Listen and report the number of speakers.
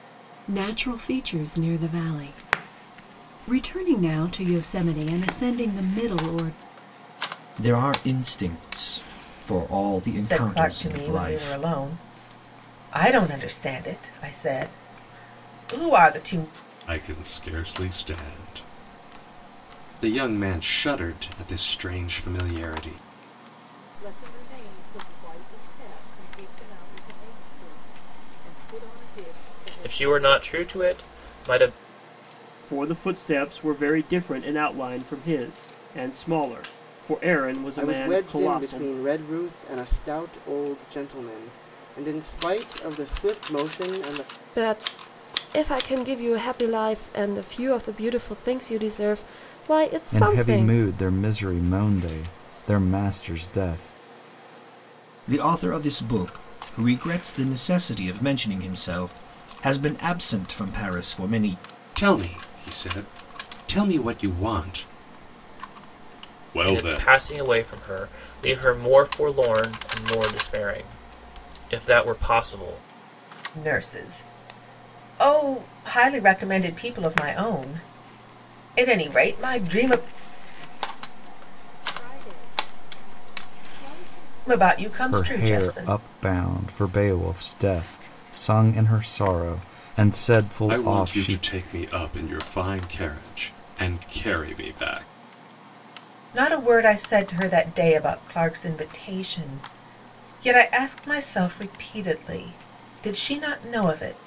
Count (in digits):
10